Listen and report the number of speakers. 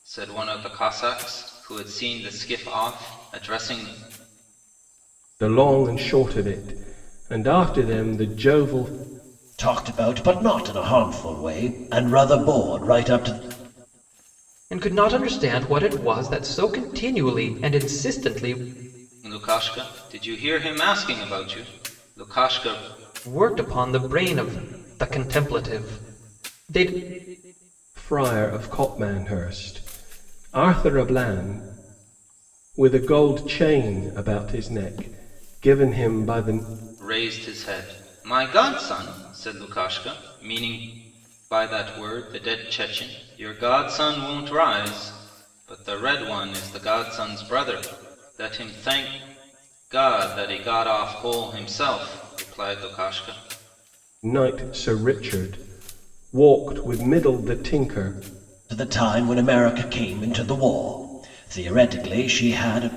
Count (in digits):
4